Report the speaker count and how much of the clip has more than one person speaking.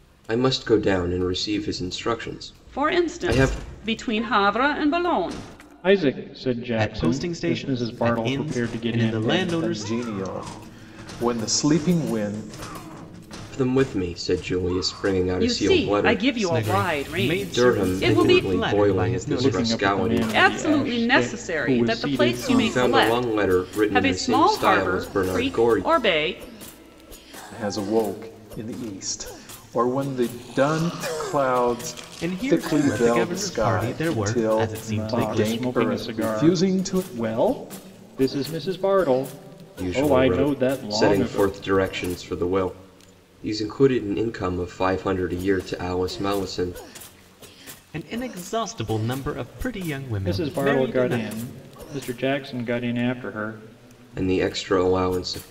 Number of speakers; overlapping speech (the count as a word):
five, about 39%